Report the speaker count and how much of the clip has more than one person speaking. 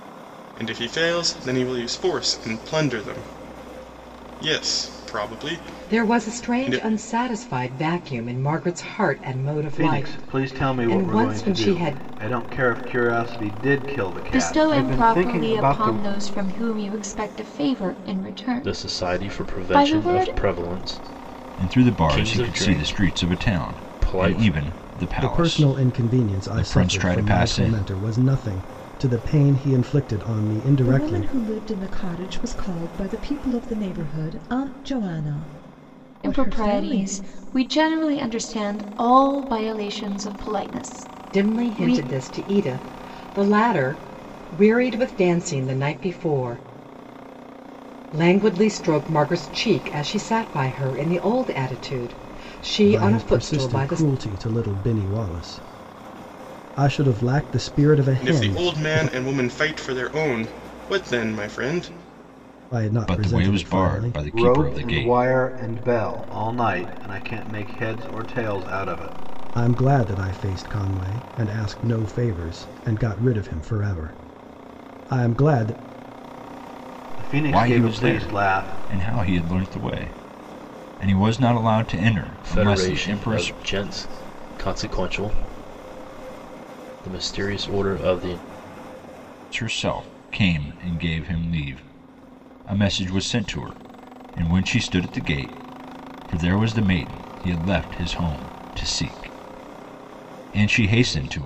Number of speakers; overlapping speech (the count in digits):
8, about 21%